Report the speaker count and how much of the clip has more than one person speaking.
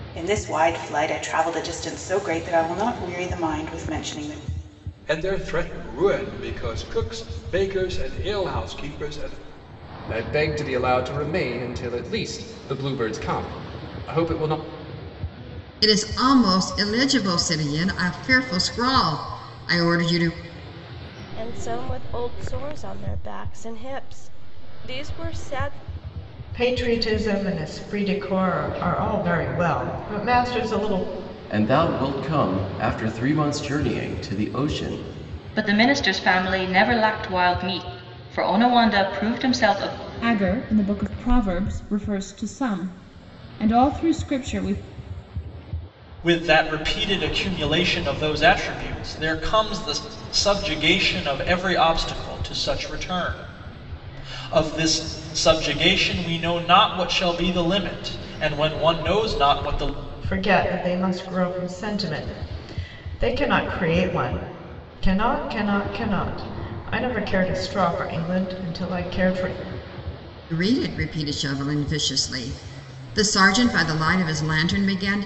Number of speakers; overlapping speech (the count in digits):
10, no overlap